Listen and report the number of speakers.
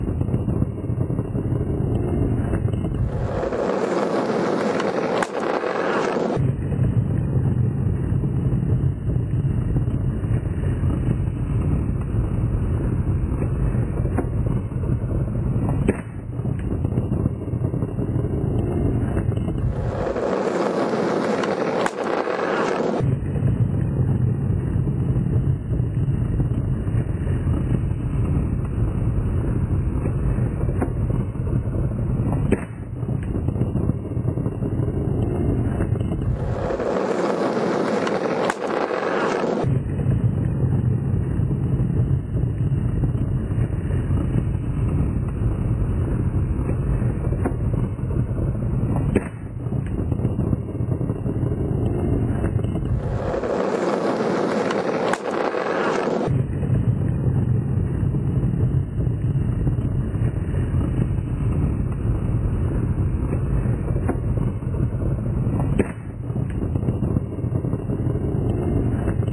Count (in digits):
0